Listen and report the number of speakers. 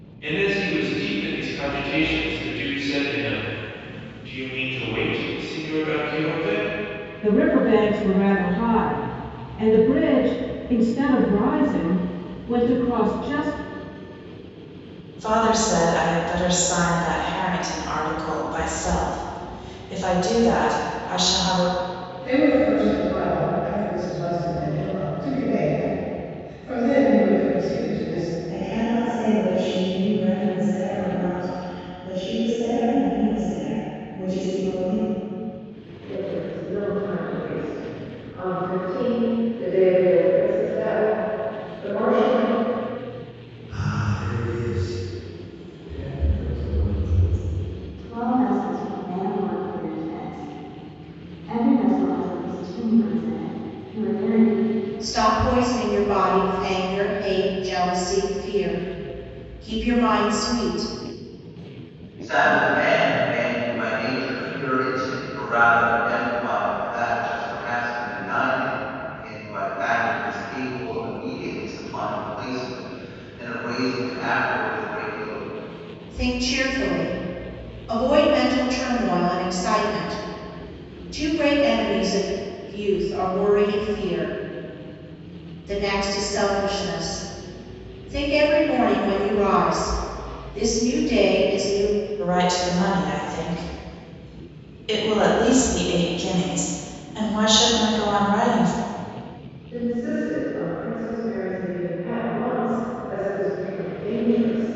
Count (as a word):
ten